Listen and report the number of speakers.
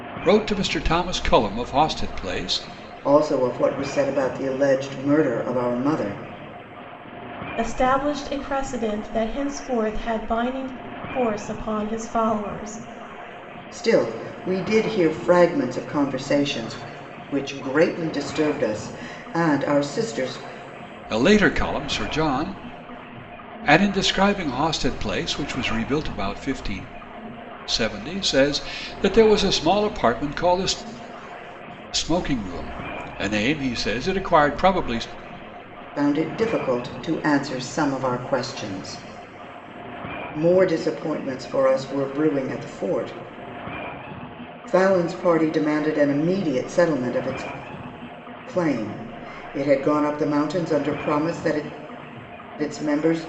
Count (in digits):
3